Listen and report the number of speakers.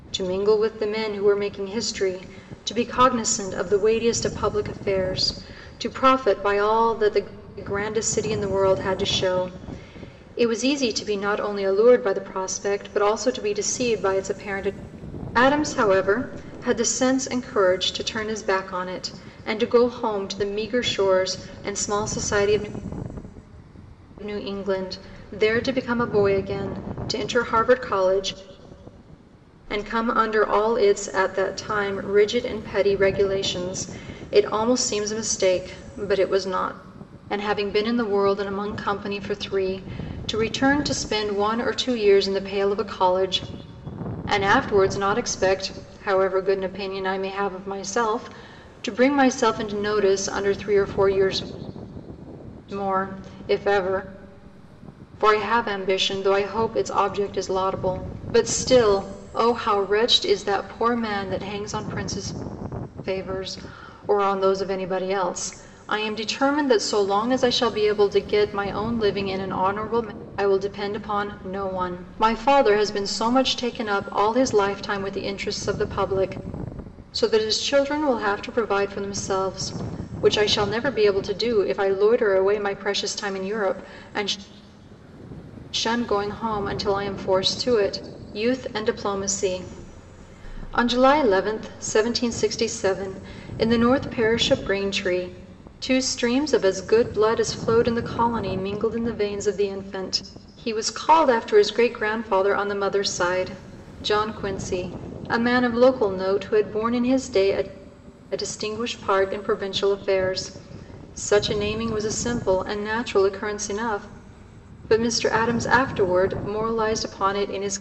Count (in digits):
1